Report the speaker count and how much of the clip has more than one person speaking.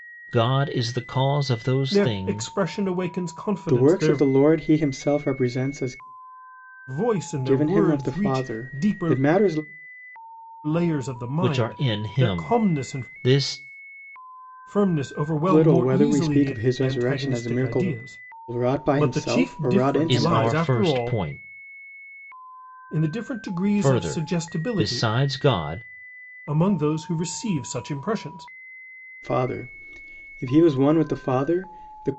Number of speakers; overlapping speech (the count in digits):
3, about 33%